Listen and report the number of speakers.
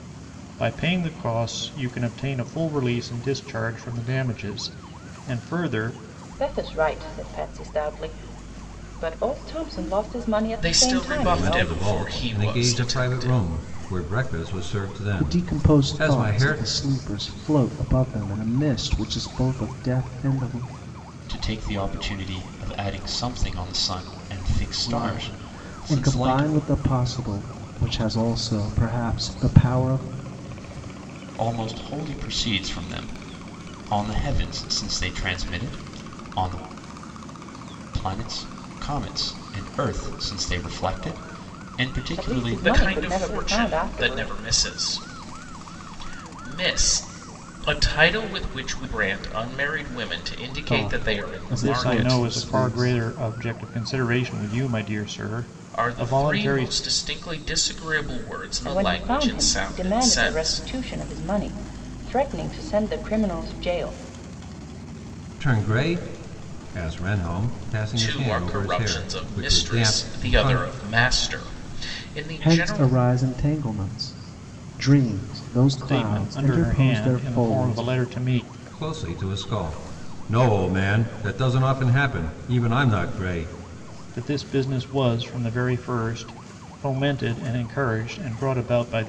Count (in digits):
6